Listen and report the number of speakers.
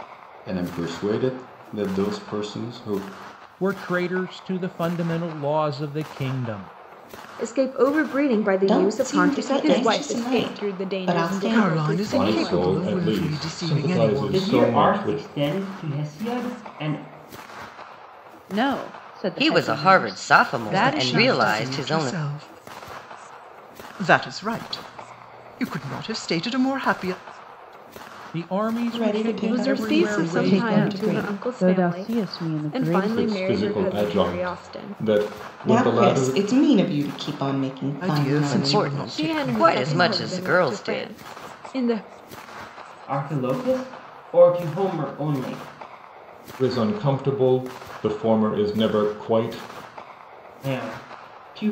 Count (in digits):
10